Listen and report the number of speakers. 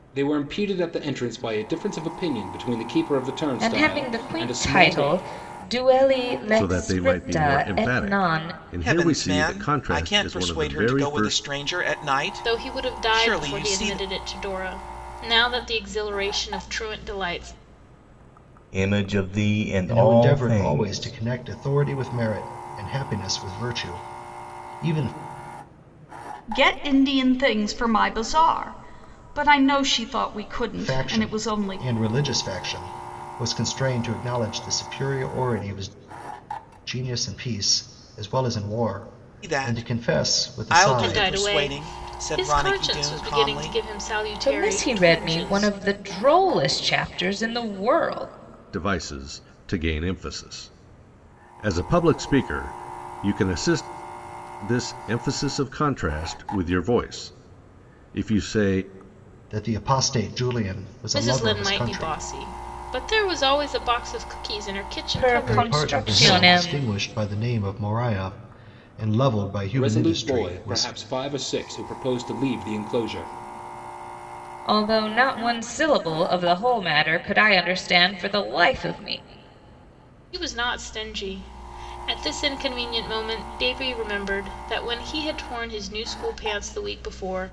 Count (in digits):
8